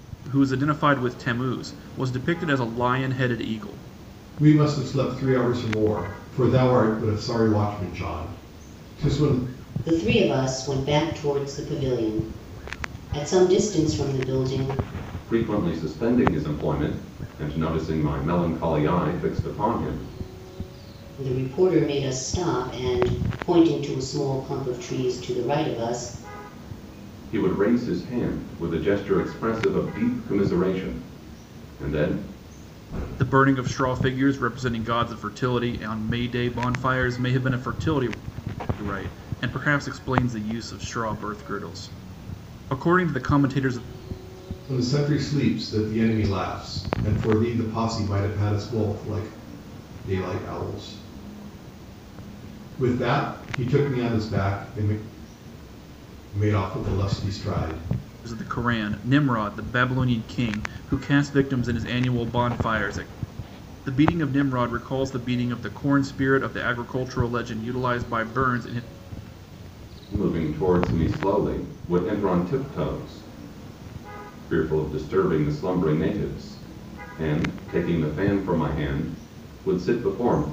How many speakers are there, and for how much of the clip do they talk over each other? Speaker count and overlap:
four, no overlap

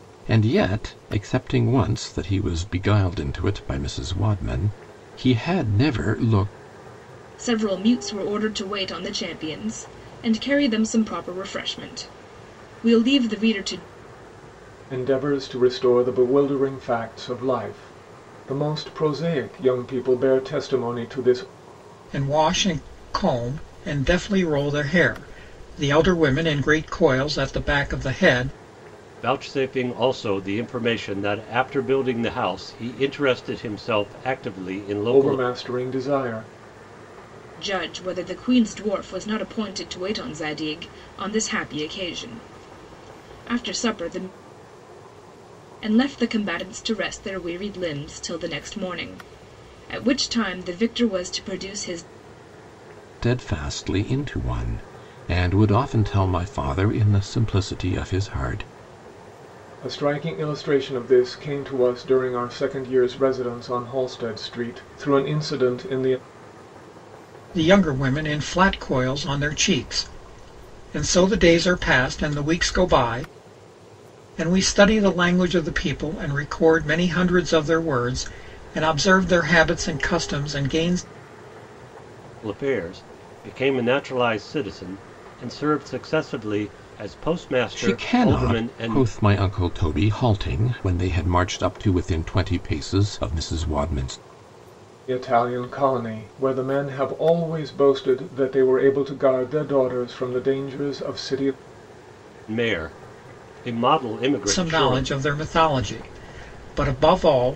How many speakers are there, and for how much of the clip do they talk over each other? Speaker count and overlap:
five, about 2%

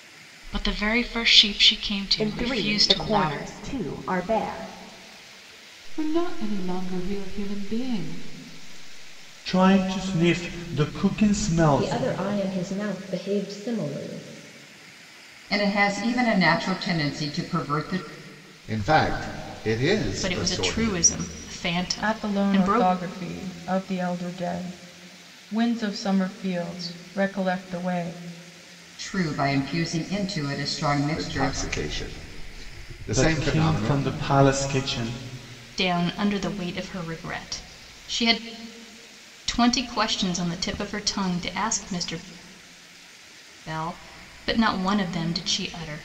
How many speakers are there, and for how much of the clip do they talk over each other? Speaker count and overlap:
nine, about 10%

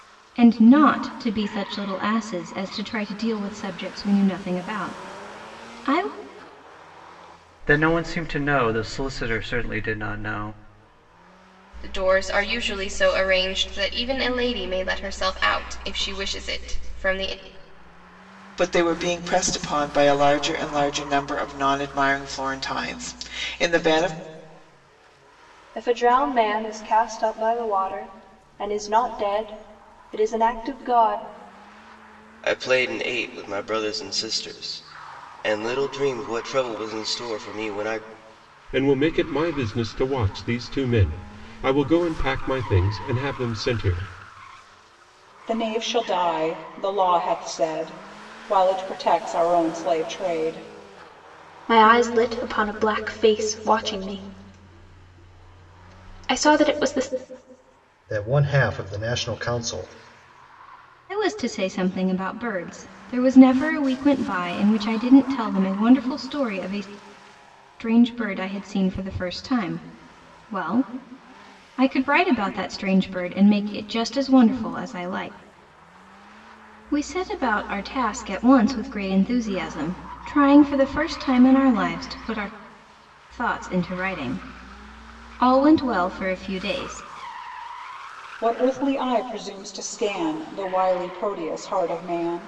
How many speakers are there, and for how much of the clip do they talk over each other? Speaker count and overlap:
ten, no overlap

